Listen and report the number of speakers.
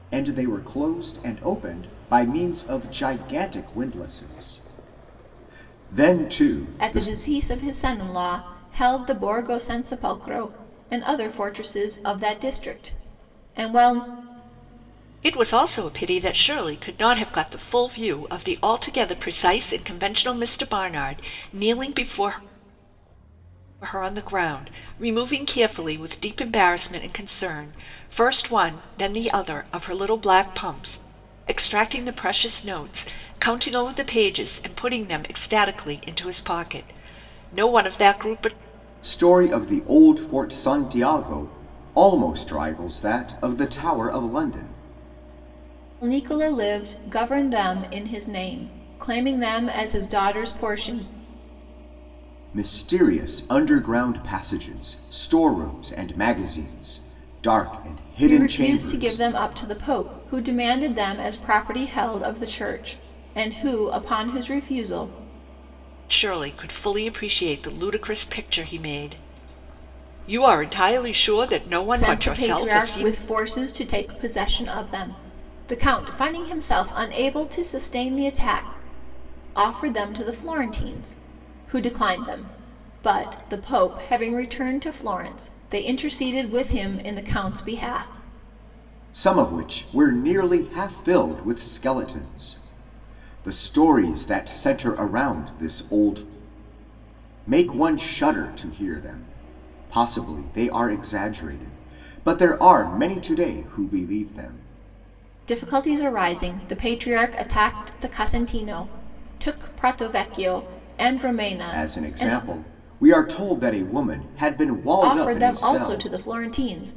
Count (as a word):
three